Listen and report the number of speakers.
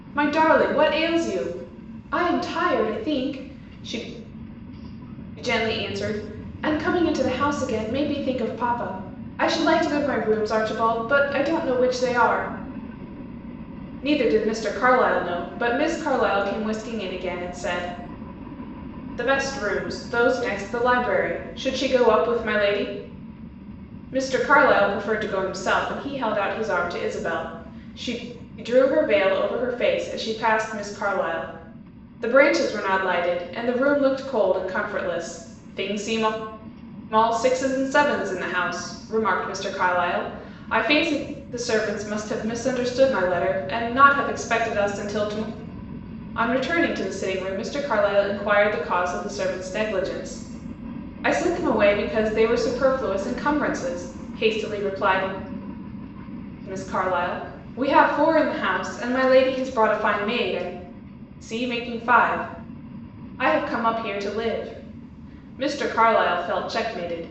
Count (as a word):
one